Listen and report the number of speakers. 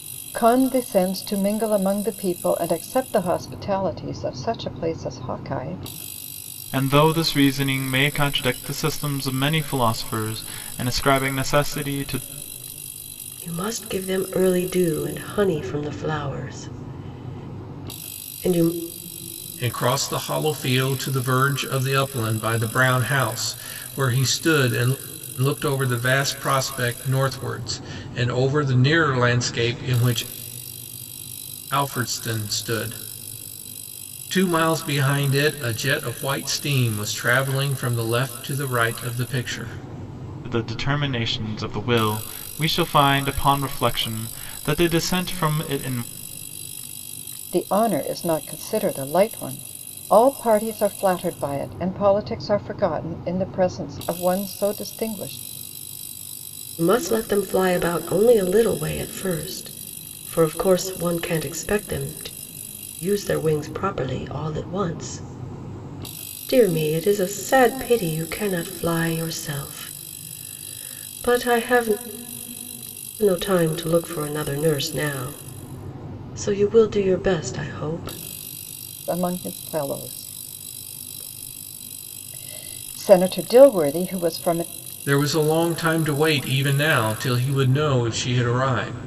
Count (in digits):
4